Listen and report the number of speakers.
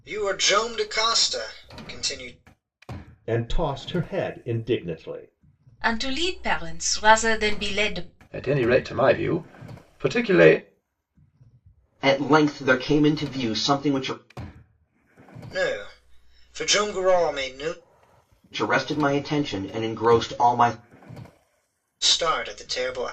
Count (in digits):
5